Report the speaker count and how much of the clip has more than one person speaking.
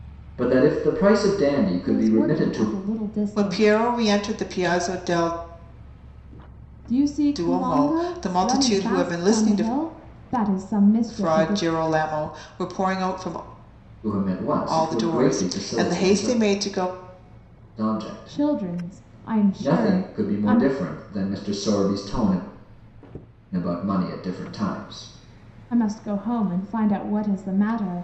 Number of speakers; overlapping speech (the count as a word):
three, about 31%